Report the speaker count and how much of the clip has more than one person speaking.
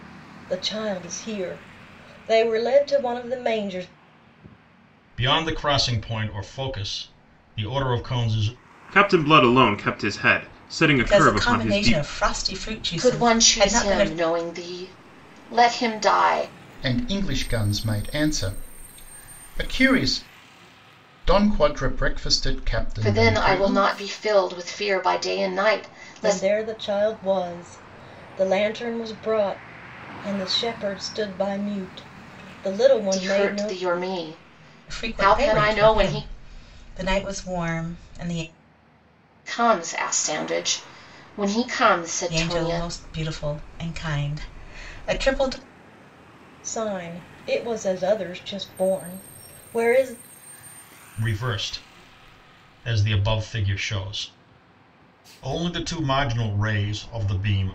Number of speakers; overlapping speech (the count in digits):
6, about 11%